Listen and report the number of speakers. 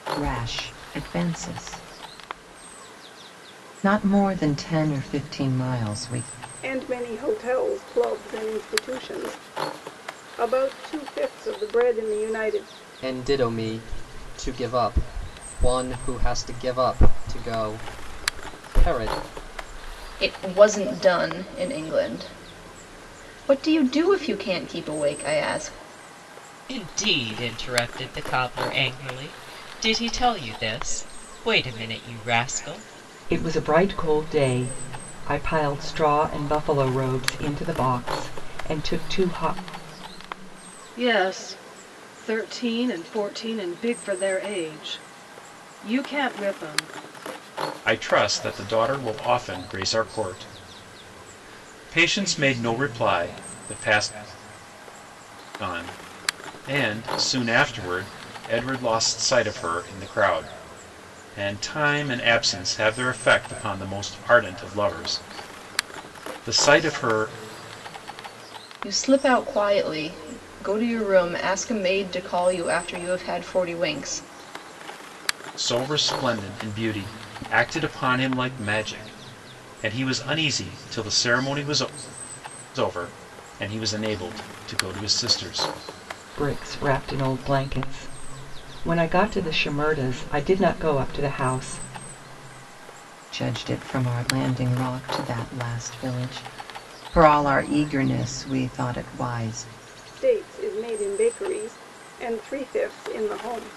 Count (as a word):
eight